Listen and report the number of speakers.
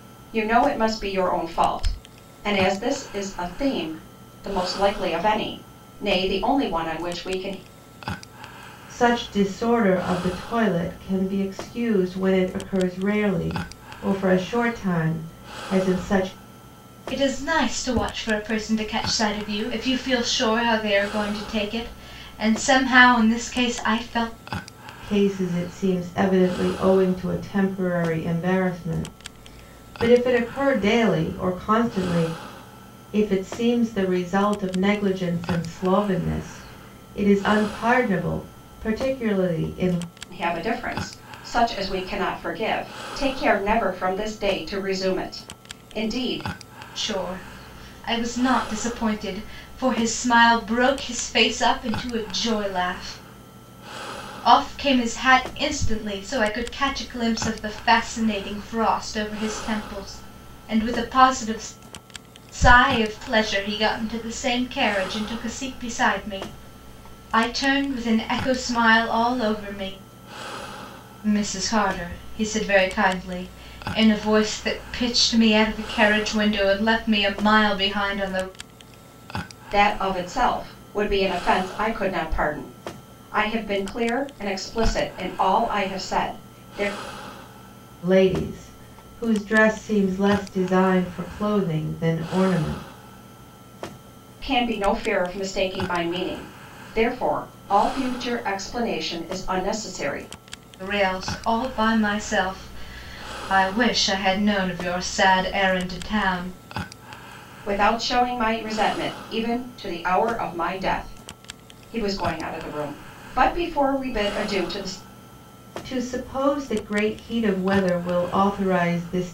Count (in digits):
3